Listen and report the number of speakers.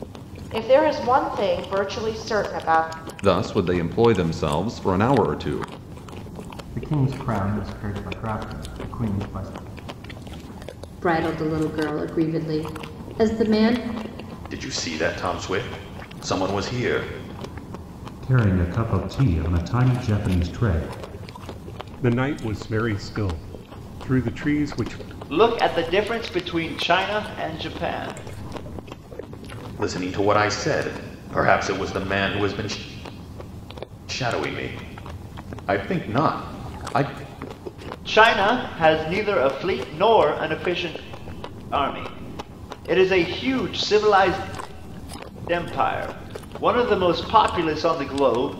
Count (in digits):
8